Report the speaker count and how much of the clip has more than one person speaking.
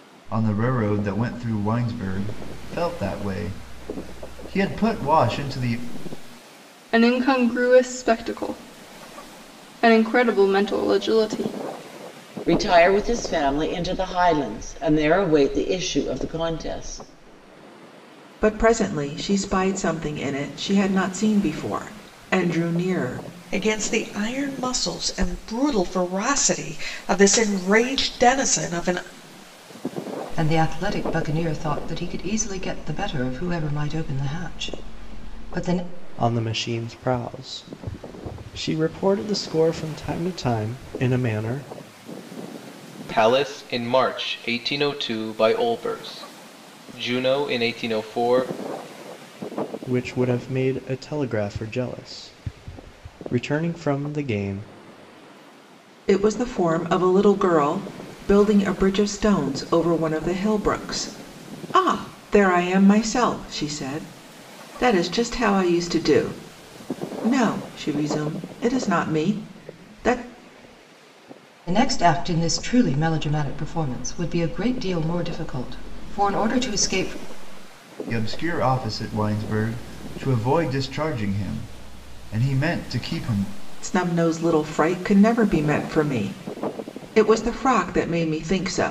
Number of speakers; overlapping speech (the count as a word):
eight, no overlap